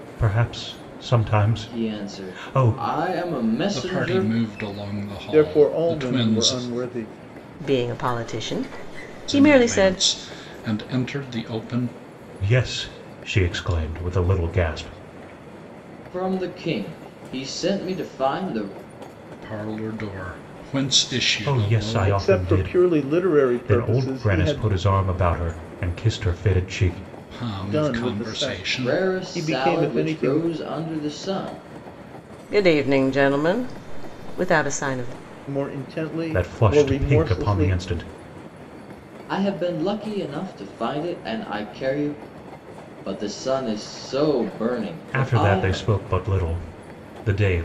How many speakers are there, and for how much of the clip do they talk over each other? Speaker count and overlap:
five, about 25%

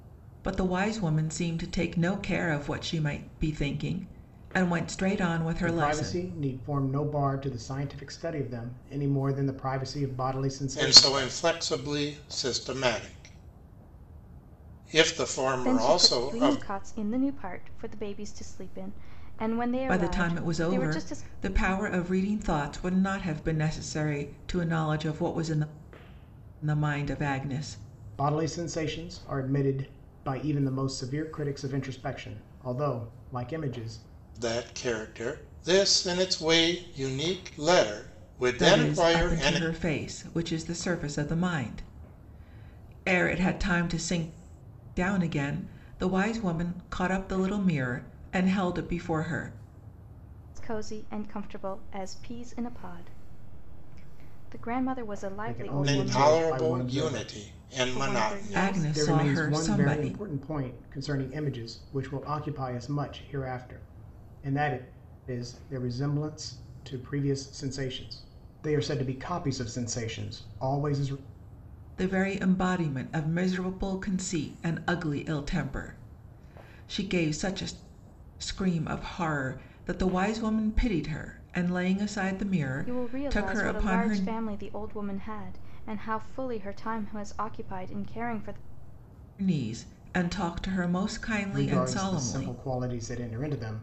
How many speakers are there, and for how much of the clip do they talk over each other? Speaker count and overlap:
four, about 13%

